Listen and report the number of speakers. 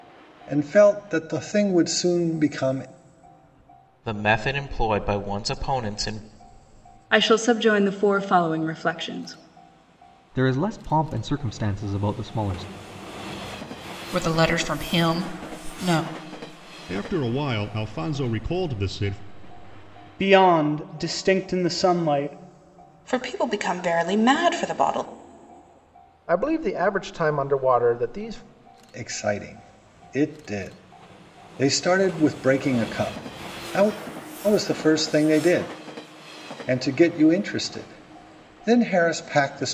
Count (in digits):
9